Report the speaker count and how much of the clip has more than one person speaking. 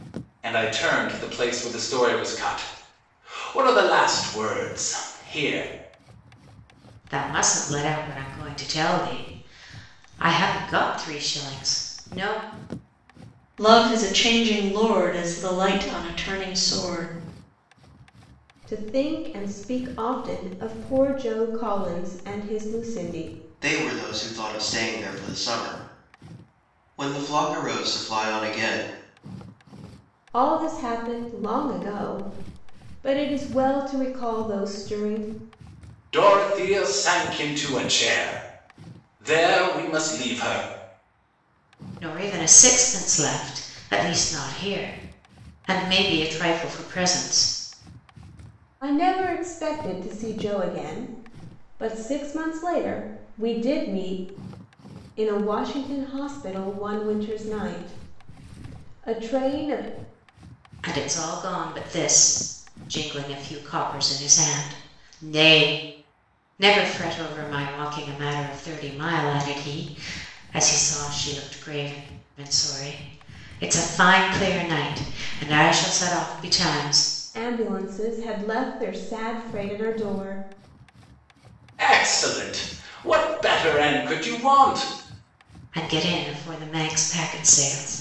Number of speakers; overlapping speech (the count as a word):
five, no overlap